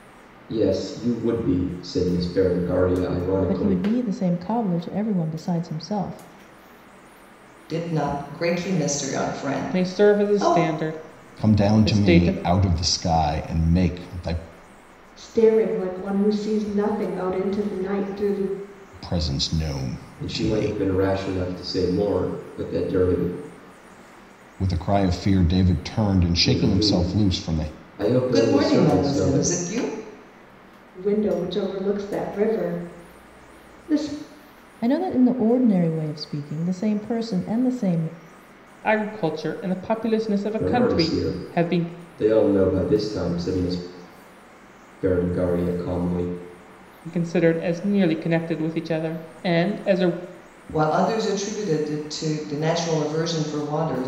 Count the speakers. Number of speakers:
6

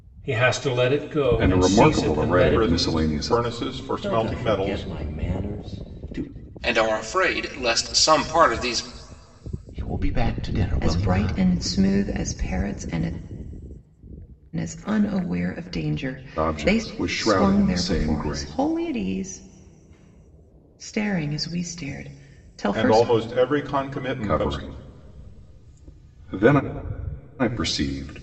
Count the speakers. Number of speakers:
7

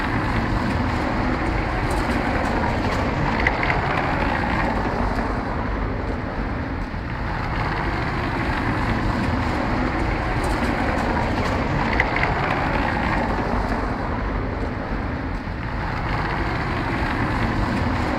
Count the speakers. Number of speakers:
0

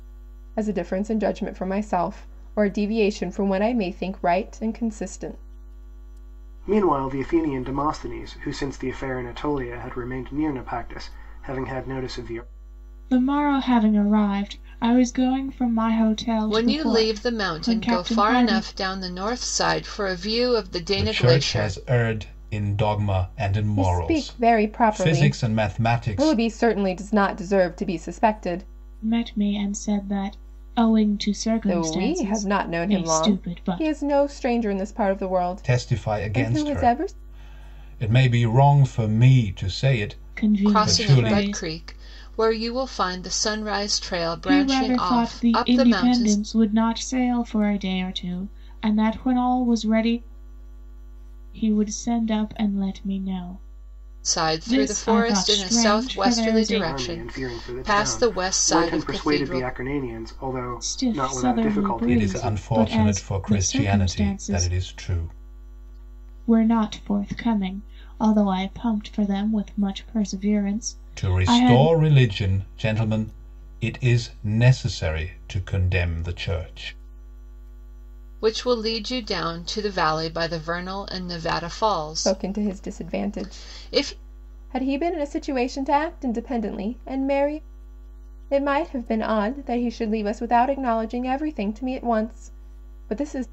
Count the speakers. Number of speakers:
5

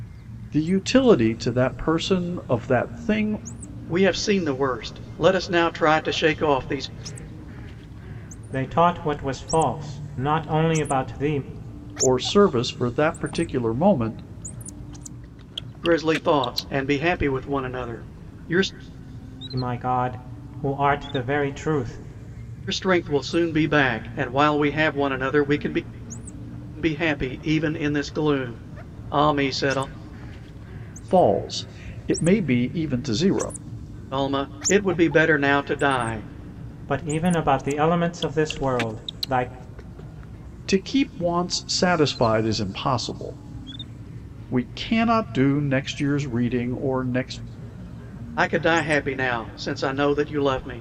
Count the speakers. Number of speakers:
3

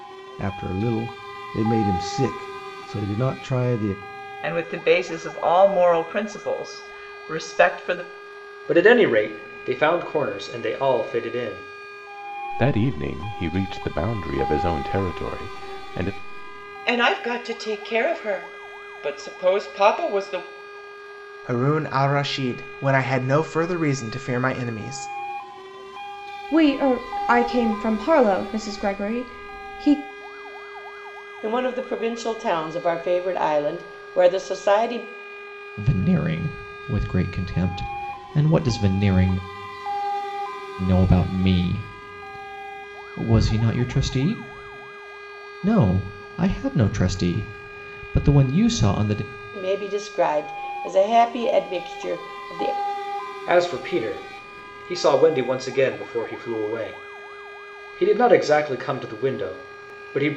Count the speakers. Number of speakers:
9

